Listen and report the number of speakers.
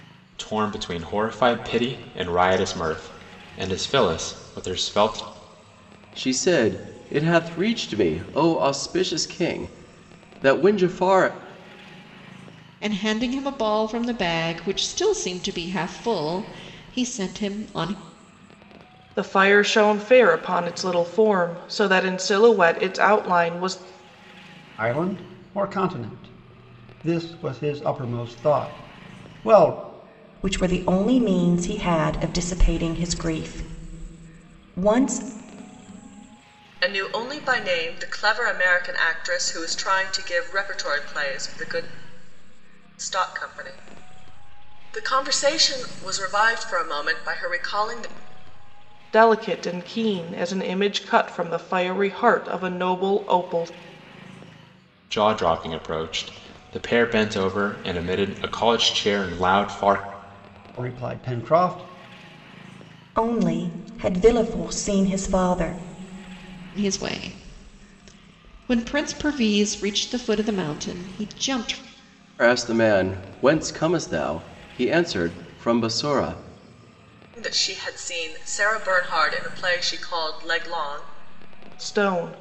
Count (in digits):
7